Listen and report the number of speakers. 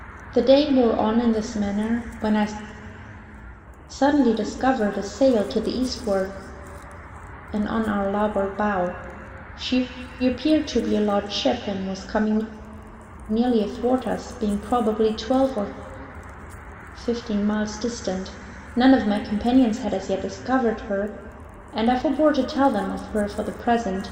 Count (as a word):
one